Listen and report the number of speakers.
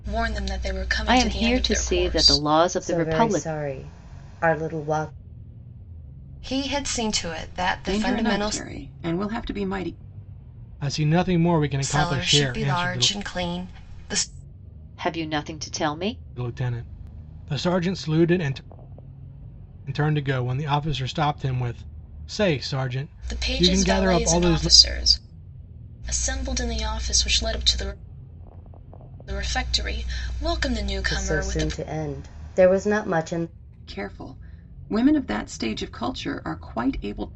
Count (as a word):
six